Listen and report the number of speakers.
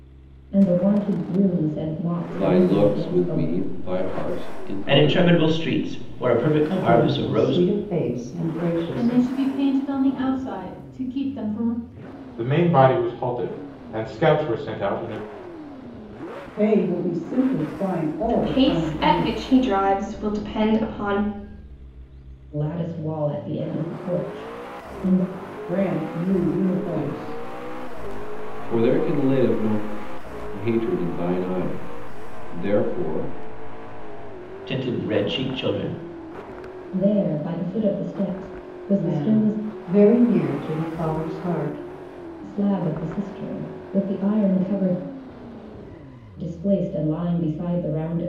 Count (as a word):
eight